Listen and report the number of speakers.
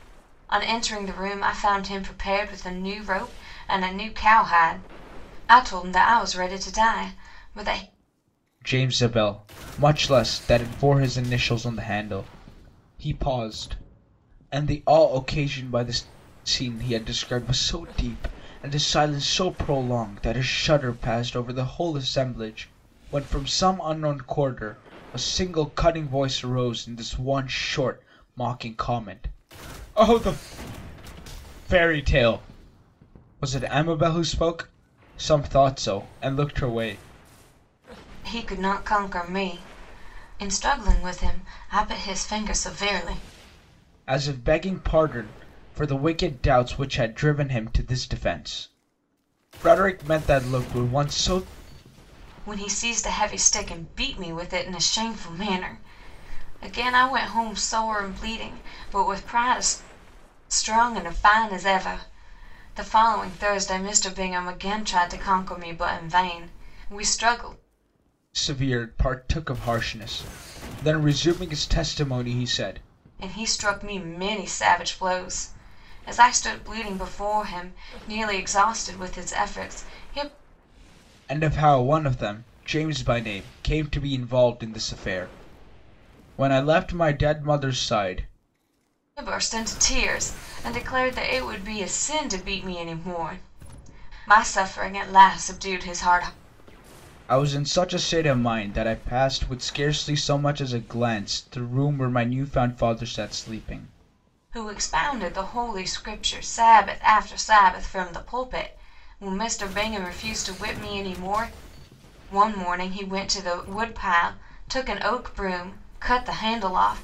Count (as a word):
two